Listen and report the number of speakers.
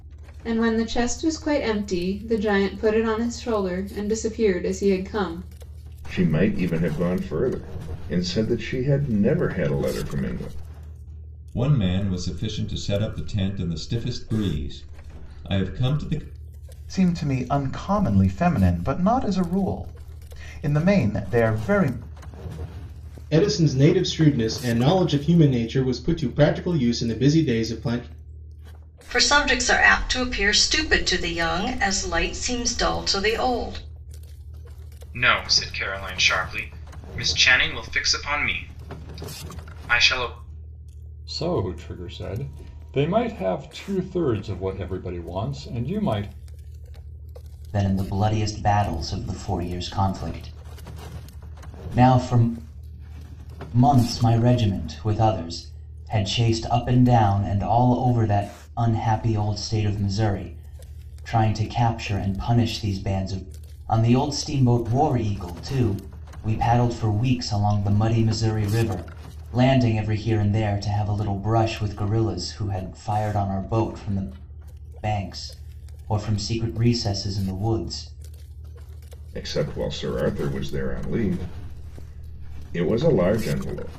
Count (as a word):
nine